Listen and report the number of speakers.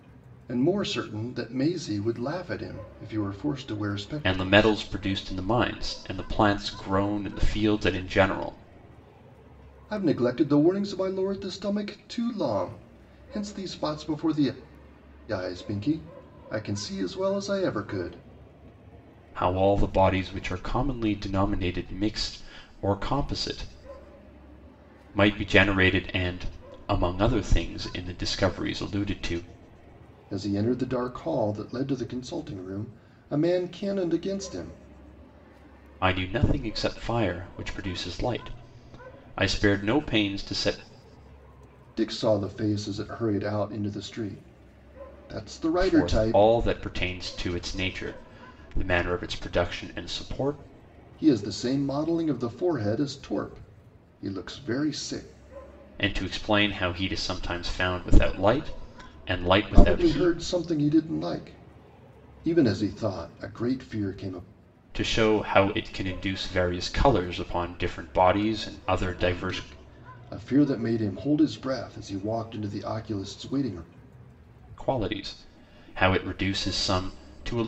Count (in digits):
2